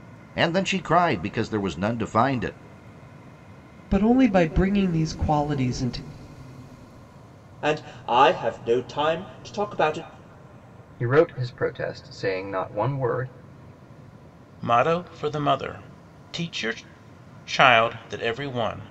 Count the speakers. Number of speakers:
five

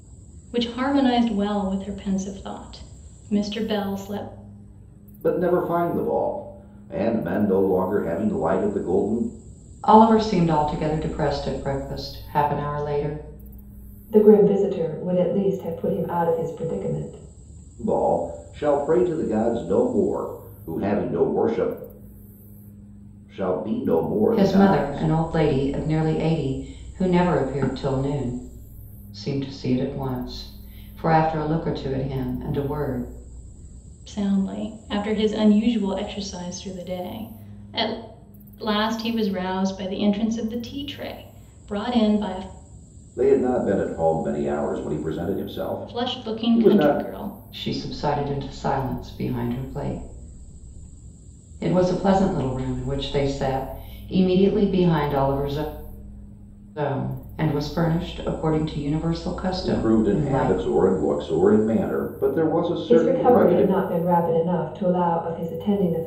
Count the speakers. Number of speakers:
four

